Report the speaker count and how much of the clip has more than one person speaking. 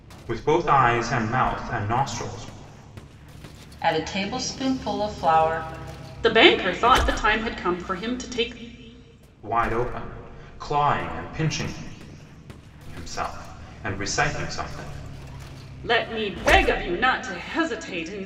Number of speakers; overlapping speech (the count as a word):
three, no overlap